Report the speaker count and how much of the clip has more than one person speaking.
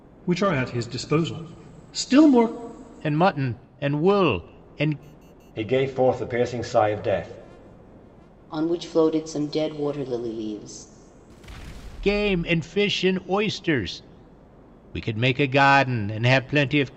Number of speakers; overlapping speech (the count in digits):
4, no overlap